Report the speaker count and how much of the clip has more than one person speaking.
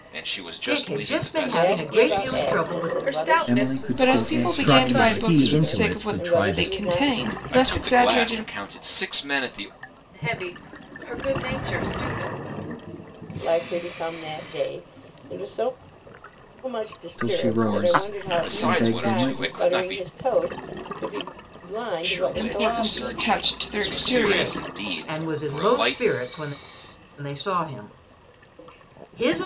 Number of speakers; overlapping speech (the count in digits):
7, about 49%